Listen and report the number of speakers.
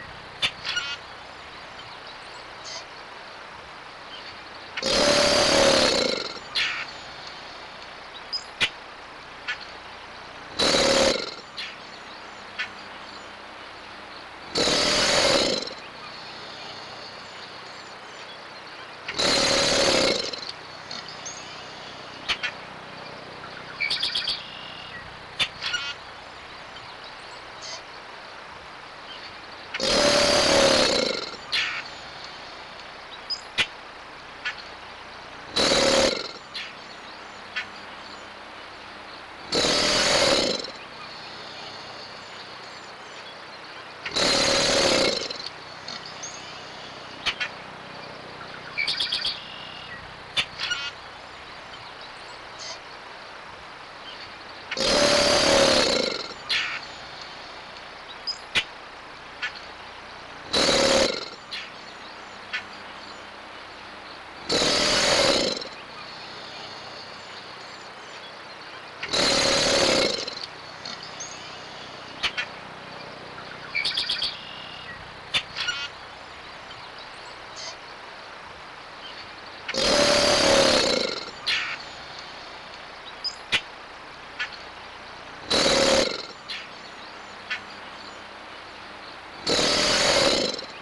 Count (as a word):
zero